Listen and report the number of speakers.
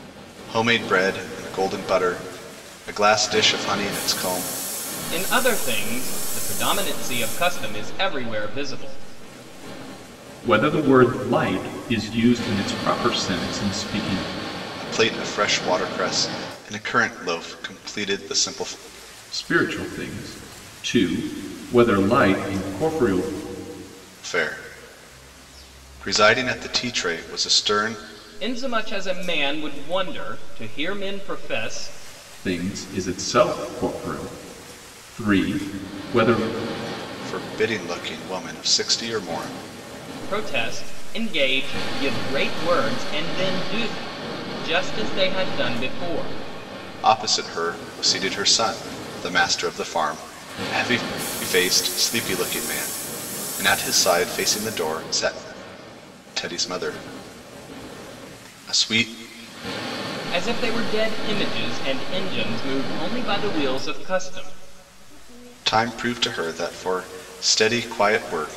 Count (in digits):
3